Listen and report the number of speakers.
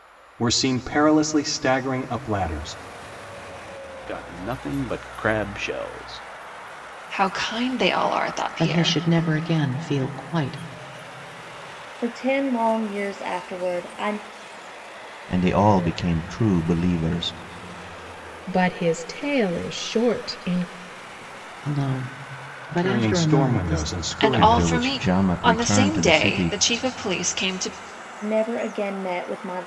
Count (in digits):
7